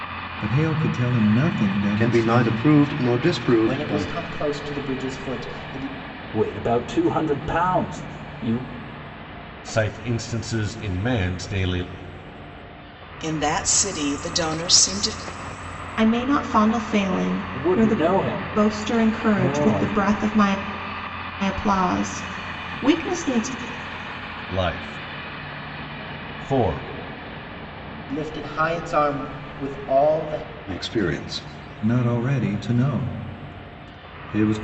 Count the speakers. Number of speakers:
7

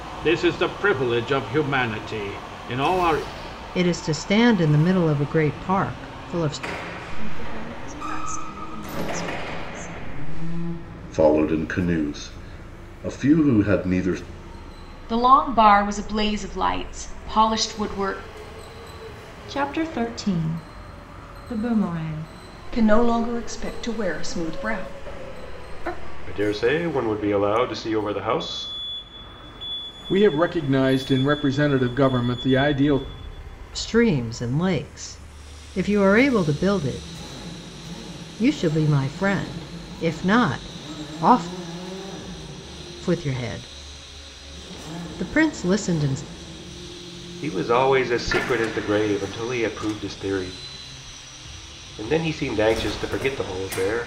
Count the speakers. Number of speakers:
9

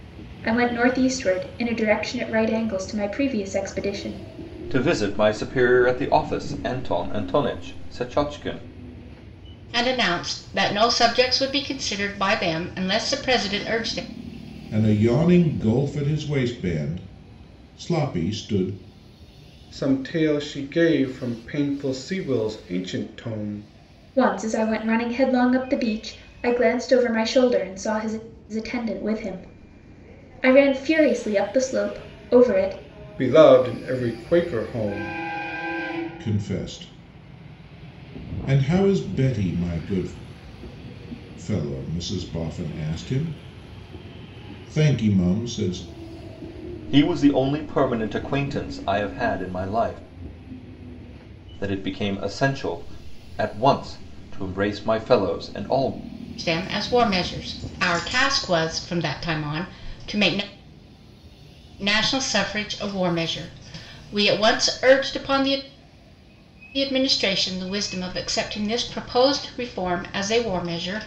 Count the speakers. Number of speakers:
5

